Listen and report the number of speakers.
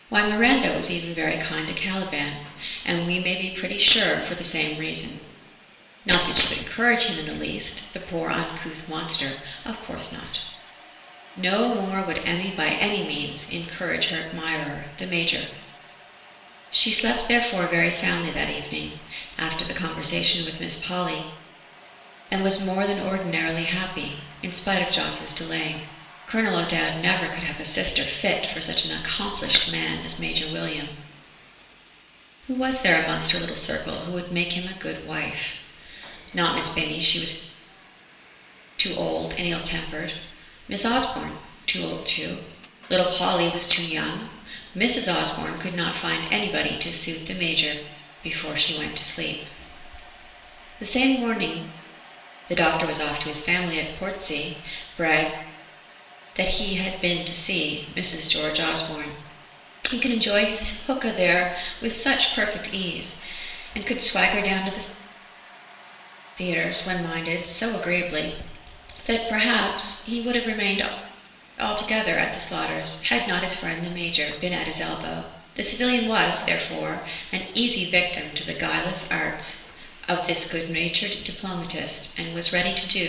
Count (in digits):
1